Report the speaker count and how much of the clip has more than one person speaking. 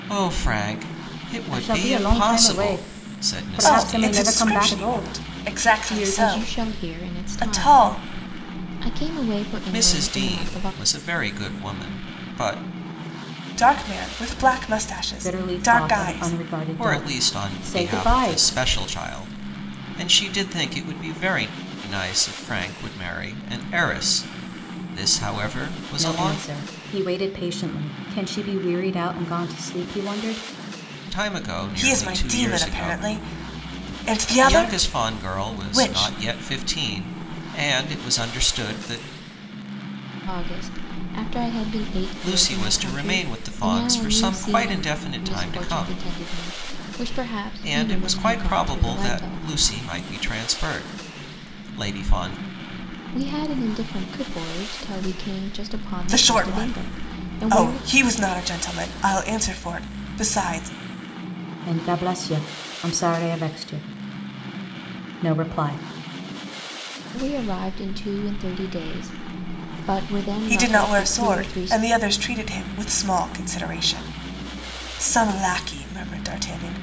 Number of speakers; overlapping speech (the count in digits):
4, about 29%